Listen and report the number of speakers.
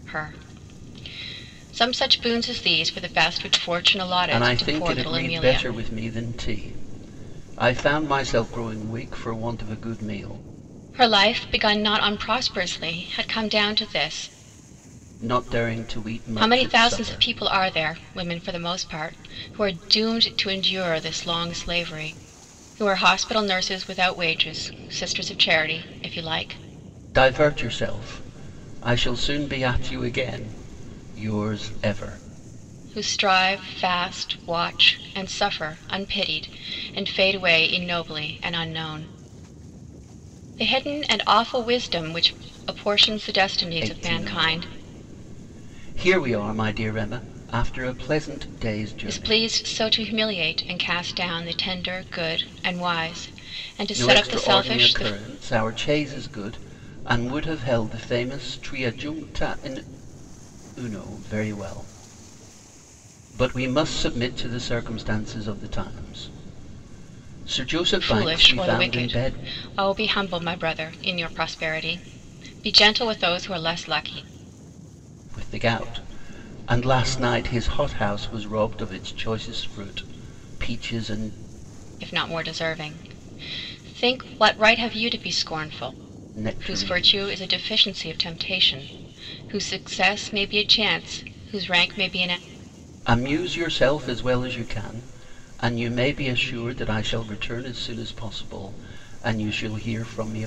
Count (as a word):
two